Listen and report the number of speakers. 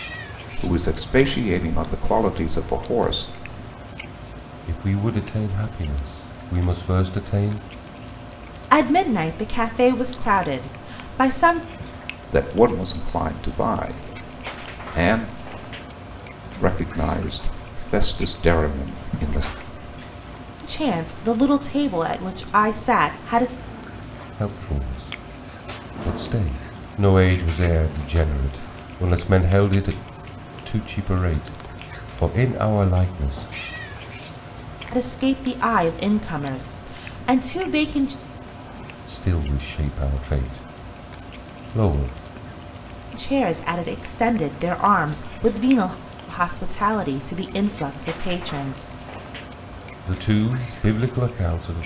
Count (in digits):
3